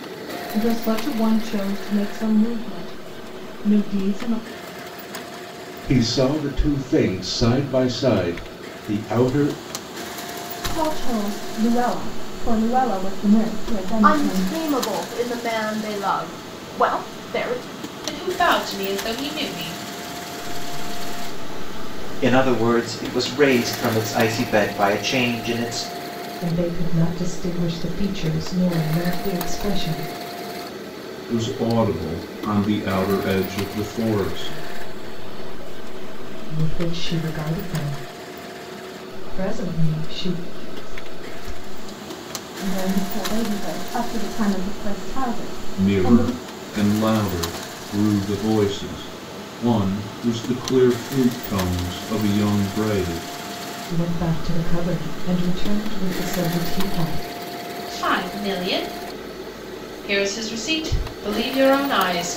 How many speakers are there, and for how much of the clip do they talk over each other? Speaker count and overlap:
nine, about 6%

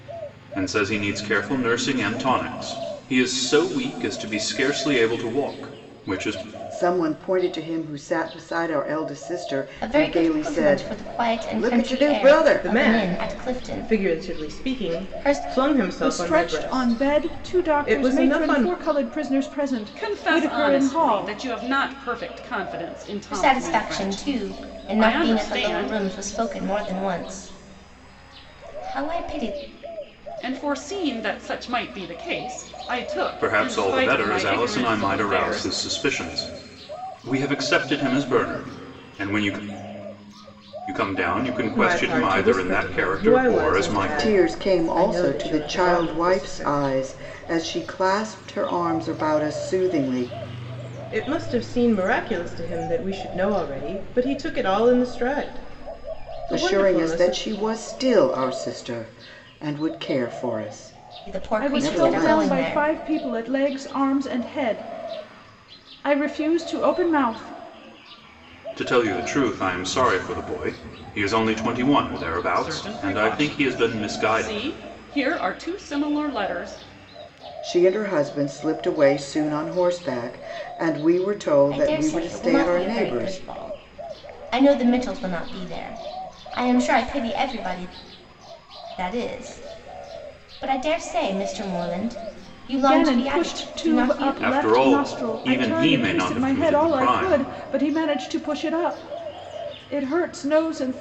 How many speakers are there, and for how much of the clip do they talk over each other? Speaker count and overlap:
six, about 31%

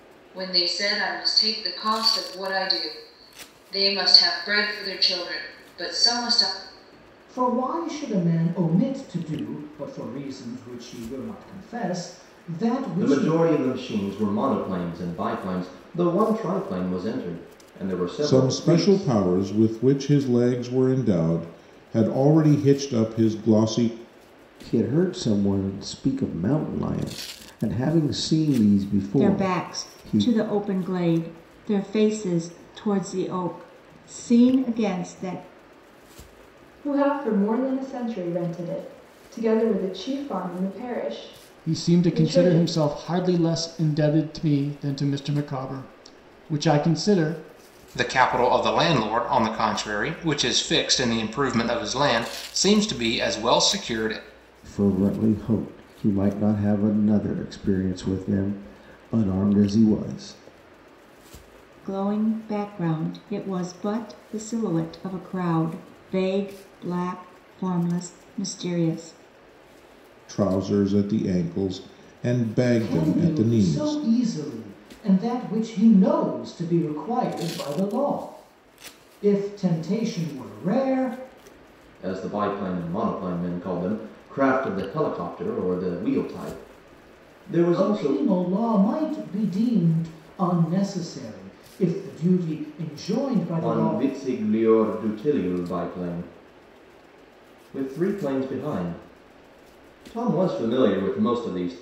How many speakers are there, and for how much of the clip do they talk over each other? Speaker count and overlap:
nine, about 6%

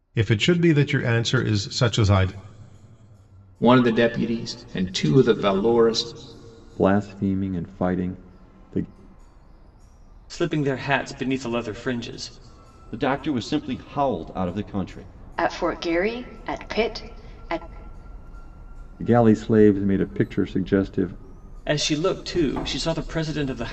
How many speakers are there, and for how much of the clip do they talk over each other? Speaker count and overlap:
six, no overlap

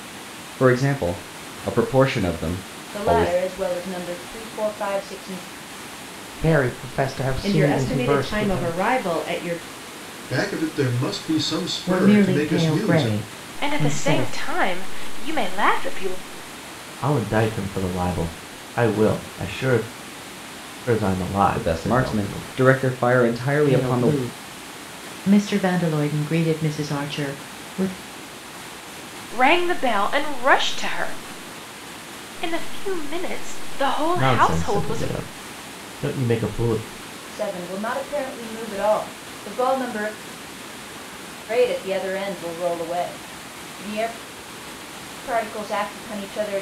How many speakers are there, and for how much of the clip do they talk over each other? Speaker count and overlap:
eight, about 14%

